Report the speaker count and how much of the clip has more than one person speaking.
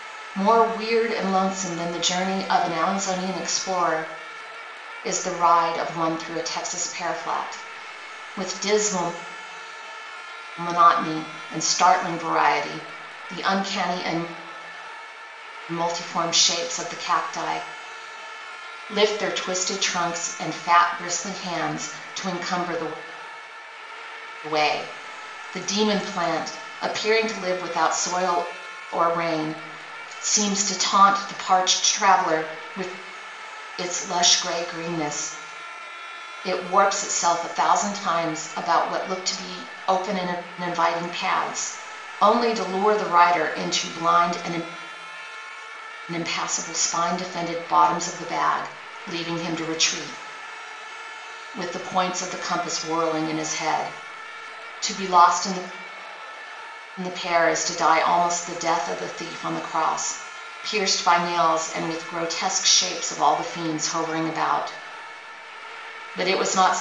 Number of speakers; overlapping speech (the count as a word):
one, no overlap